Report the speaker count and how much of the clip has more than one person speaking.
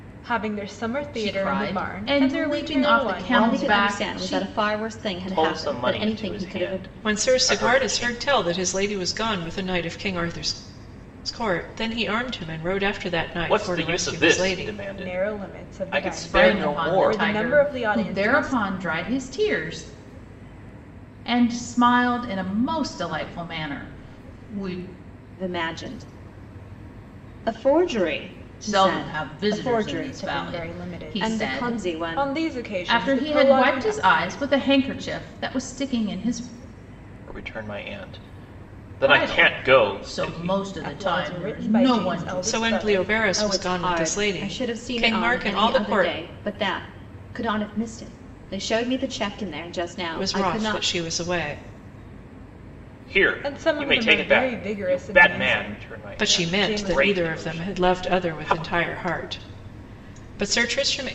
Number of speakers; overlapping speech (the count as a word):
five, about 46%